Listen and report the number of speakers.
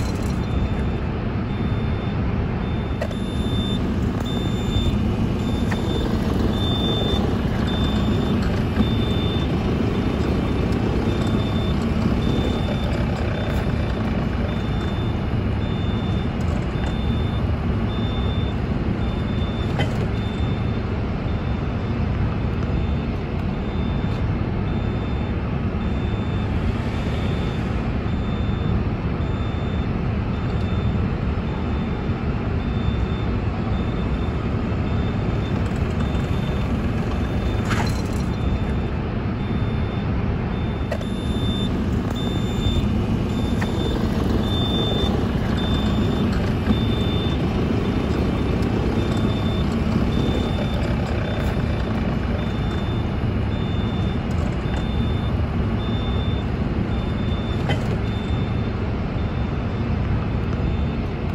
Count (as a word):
zero